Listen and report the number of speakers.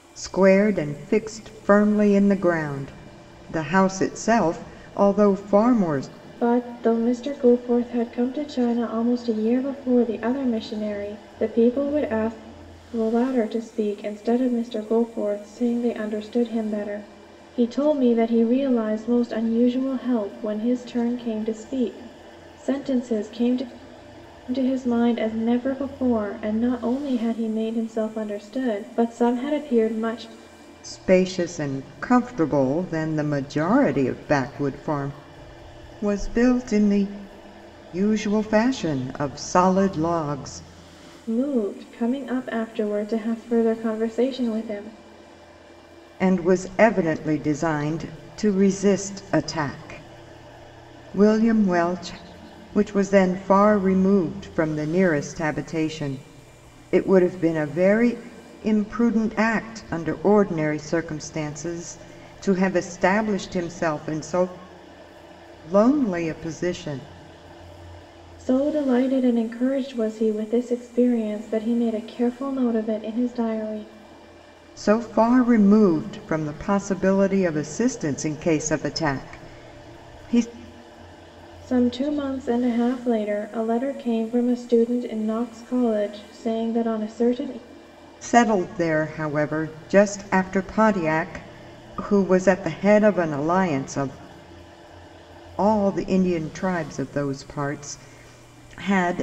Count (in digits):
2